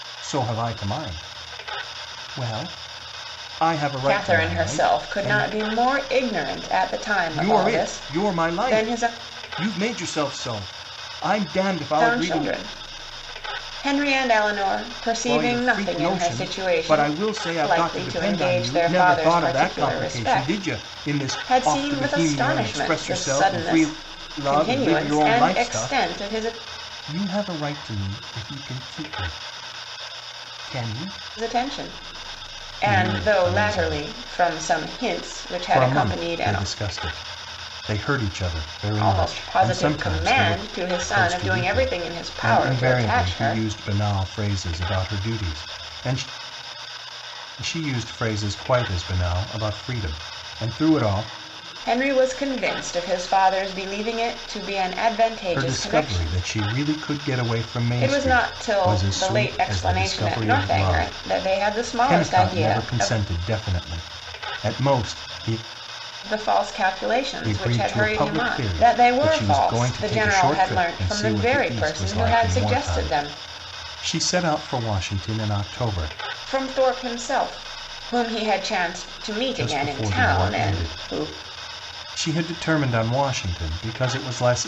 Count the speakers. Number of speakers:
2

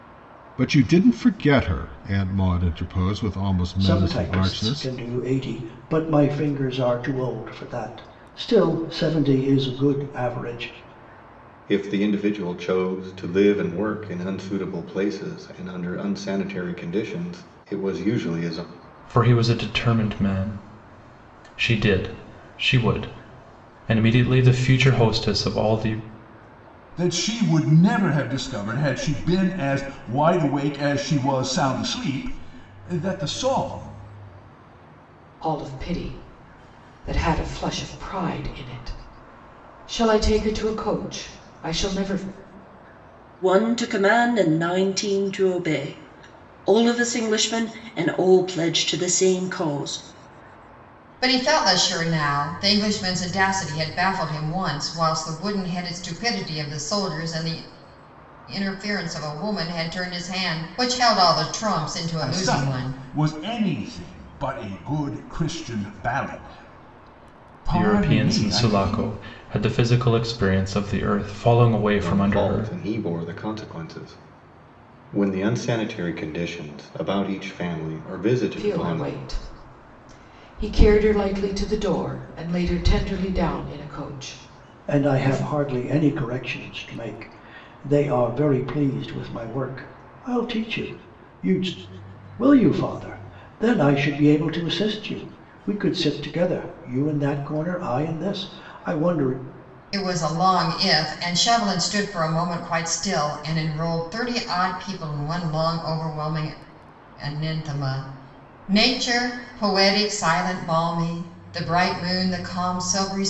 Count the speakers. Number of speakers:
8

